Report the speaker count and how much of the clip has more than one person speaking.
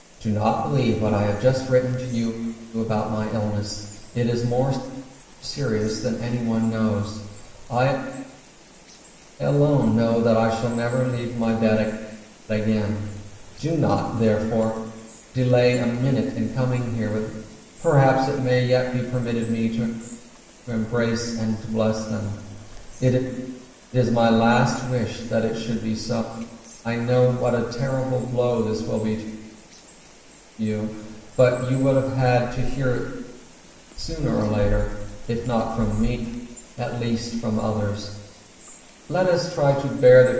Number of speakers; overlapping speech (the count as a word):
one, no overlap